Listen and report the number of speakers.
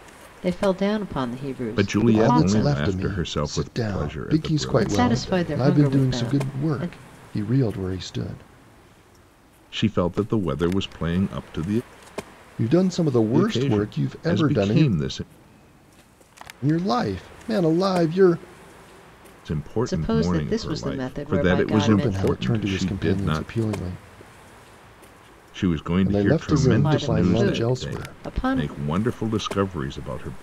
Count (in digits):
3